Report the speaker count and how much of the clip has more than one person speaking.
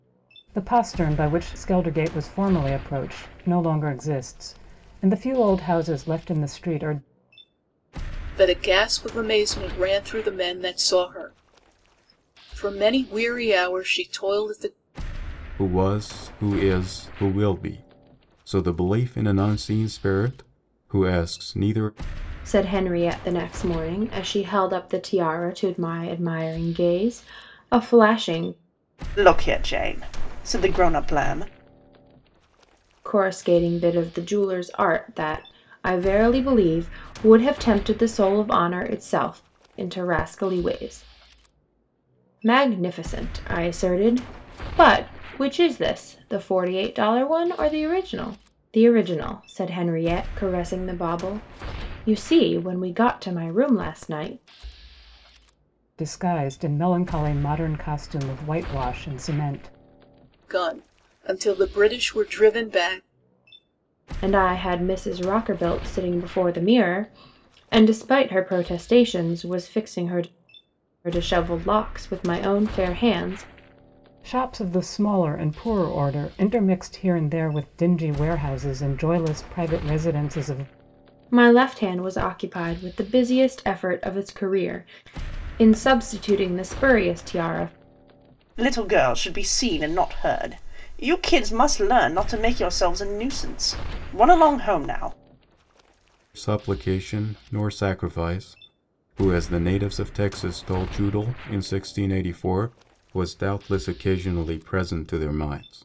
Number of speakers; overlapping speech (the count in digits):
5, no overlap